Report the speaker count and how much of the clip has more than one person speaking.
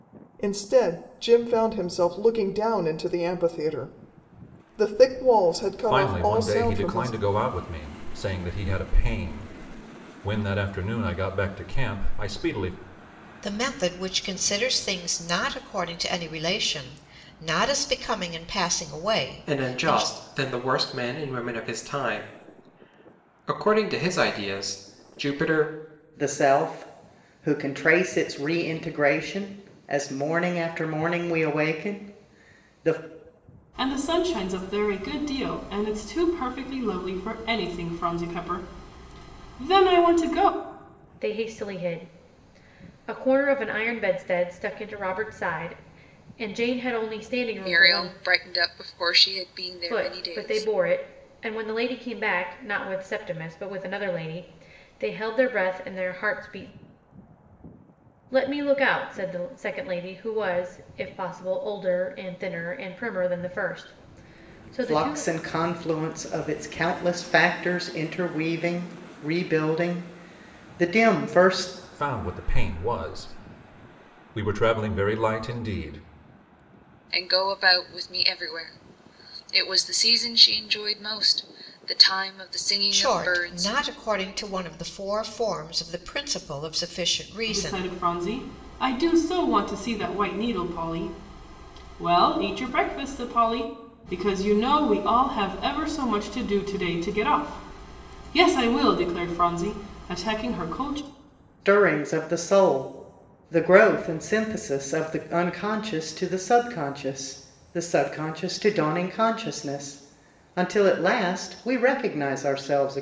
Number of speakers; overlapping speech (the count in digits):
8, about 5%